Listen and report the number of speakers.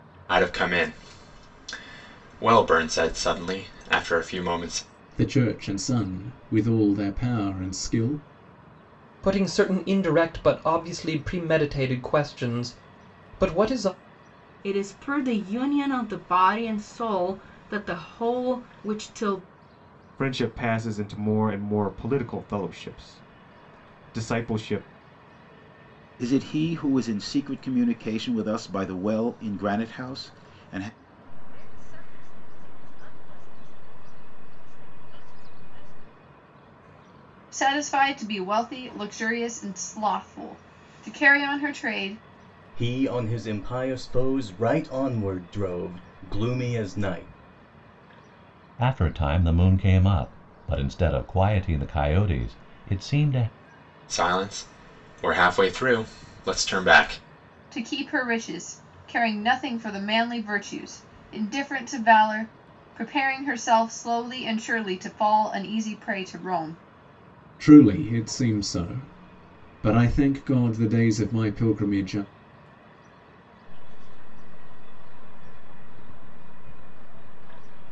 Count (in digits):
10